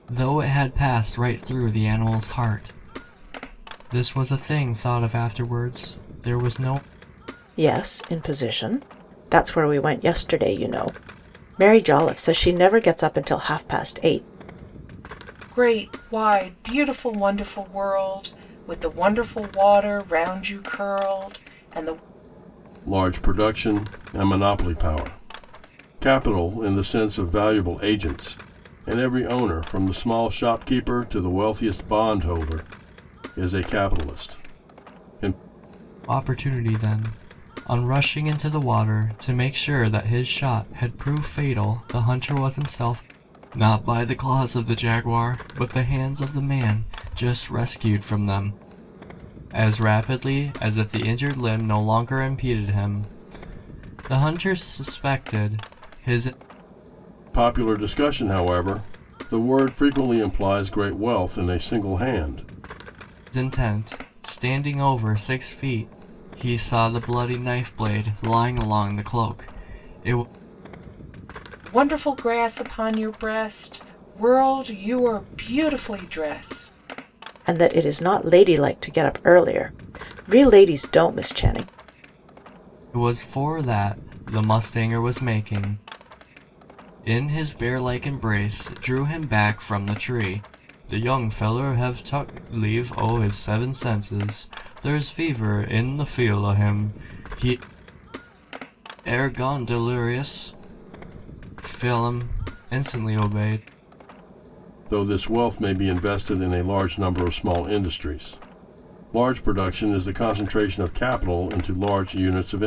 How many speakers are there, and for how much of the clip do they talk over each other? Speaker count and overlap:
four, no overlap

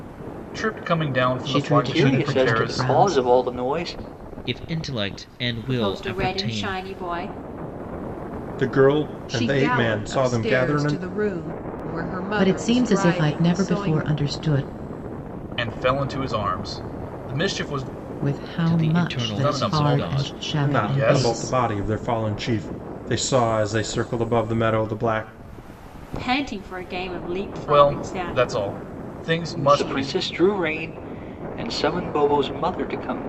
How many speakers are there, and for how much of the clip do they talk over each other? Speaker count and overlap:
seven, about 33%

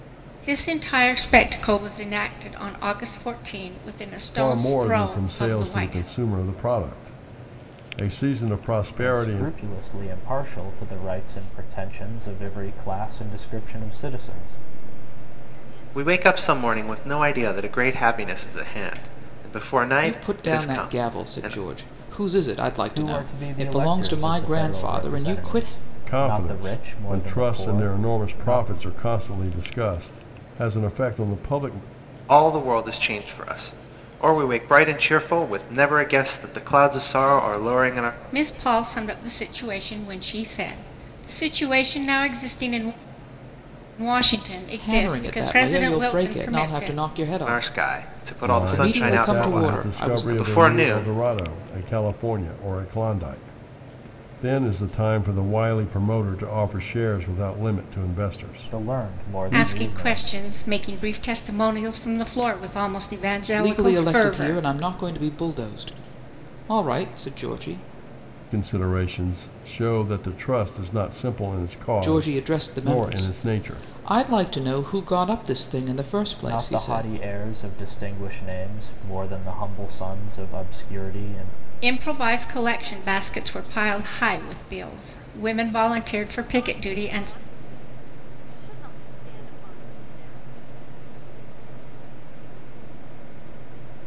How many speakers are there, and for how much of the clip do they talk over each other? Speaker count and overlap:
six, about 34%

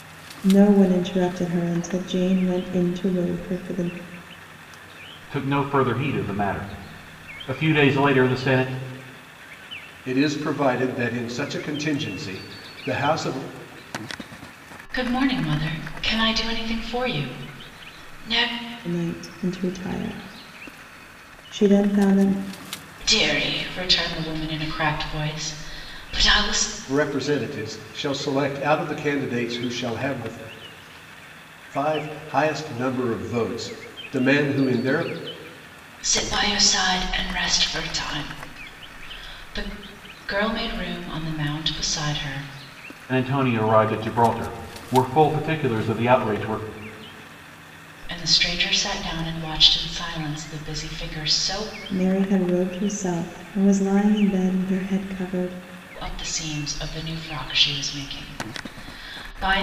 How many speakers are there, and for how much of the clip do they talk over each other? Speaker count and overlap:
four, no overlap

